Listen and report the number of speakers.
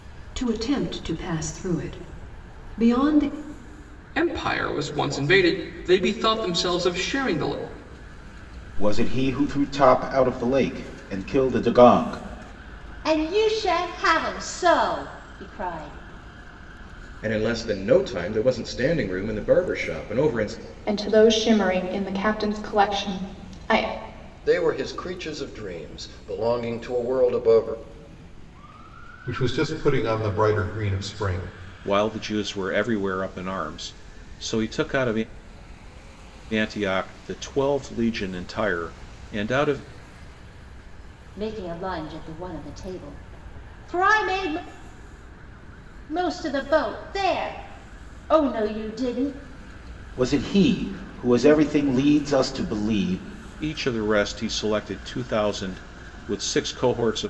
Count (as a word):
nine